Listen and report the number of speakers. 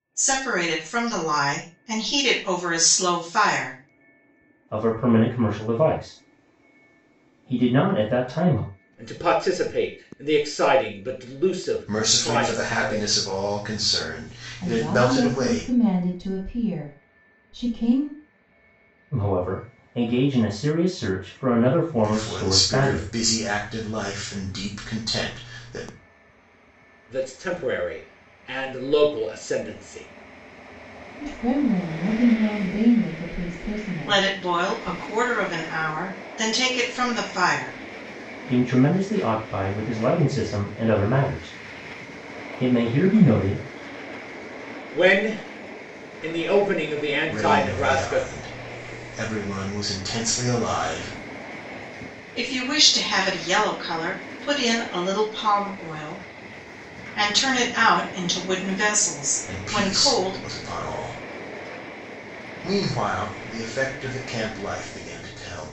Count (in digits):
5